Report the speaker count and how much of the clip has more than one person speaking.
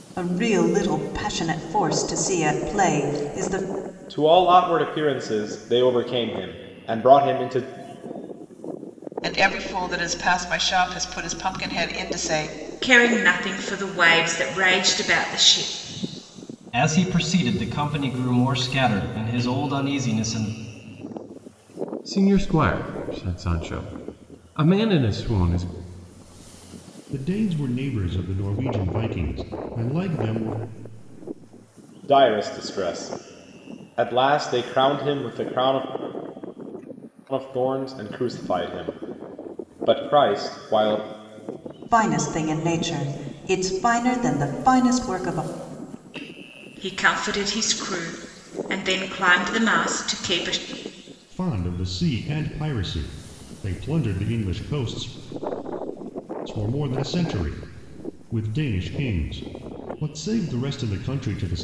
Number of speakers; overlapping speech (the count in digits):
7, no overlap